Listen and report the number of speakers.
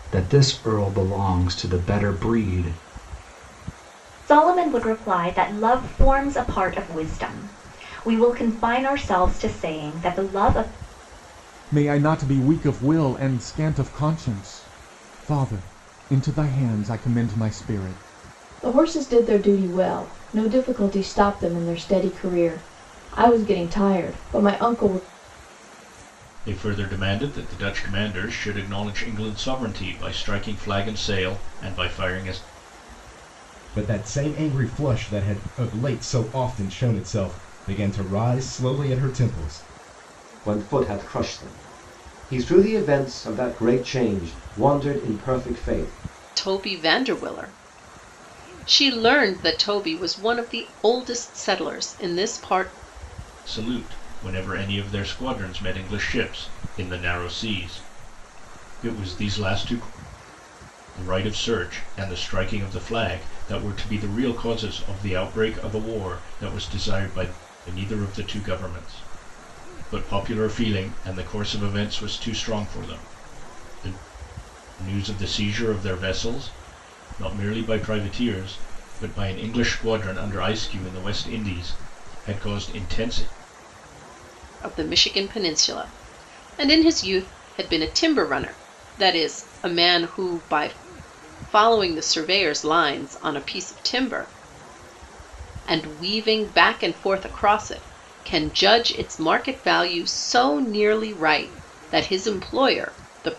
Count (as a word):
eight